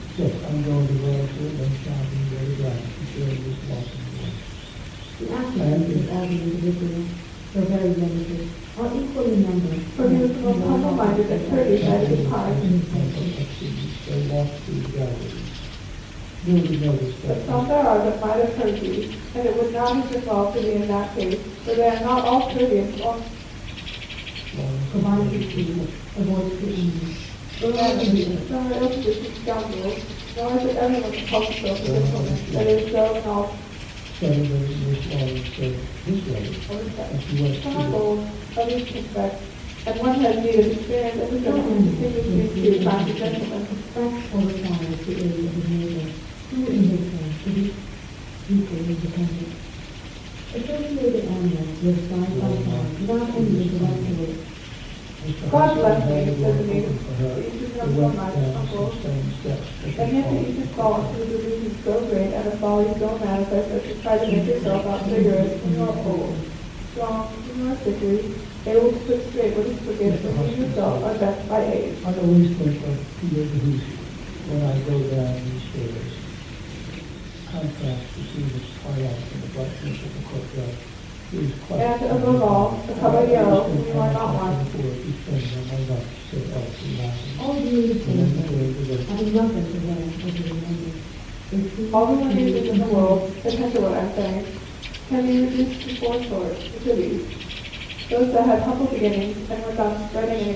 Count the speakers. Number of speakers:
three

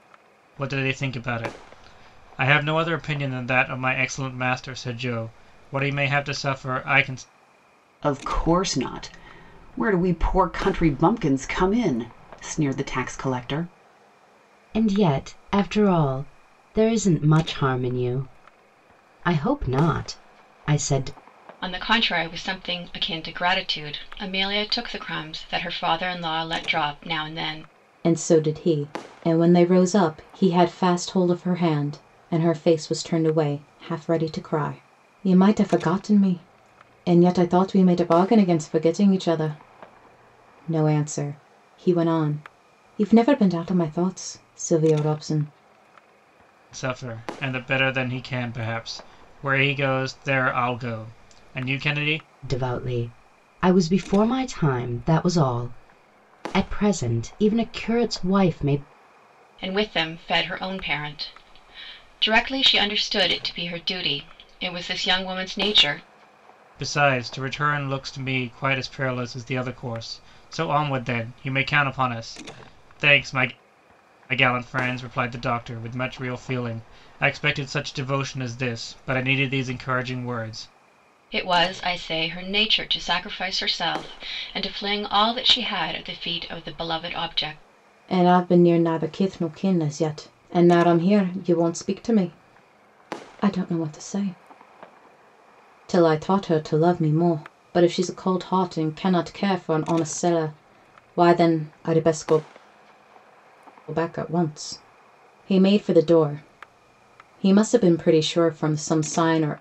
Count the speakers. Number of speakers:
five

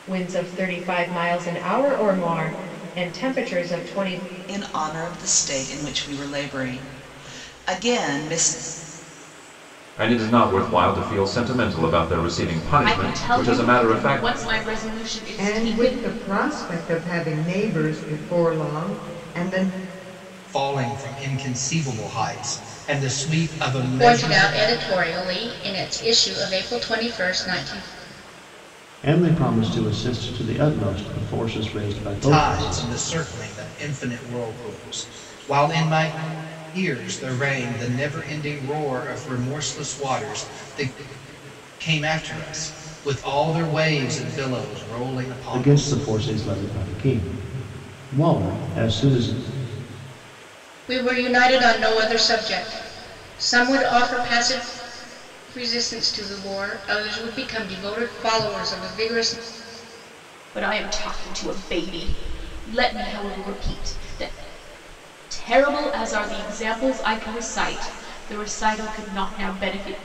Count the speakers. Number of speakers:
eight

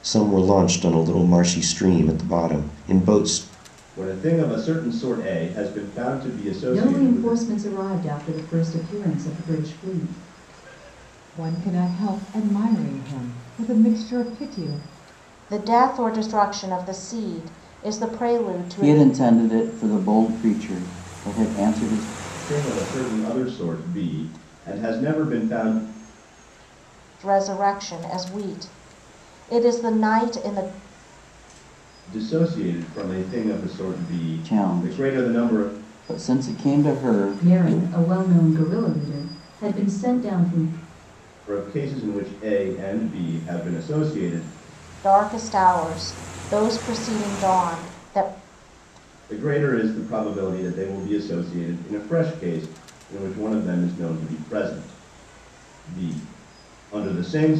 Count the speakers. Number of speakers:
six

